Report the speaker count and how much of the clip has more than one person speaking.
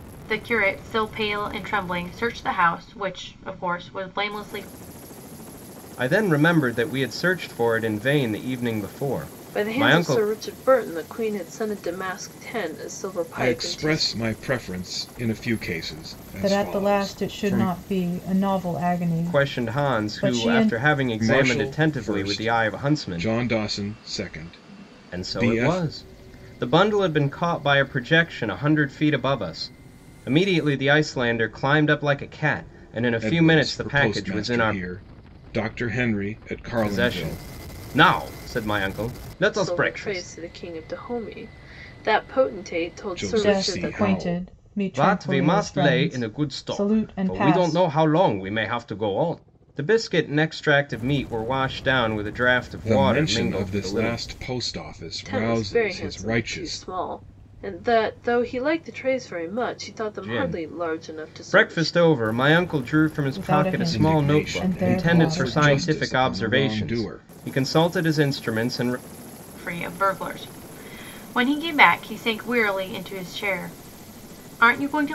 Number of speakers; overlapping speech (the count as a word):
five, about 31%